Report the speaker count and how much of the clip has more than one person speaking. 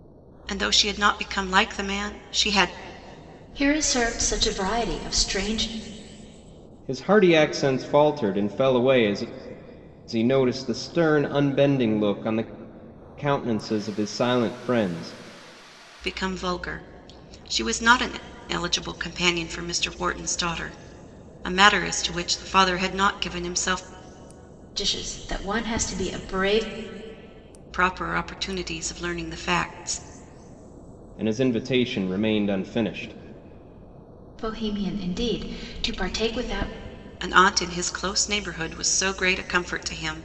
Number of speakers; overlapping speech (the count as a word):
three, no overlap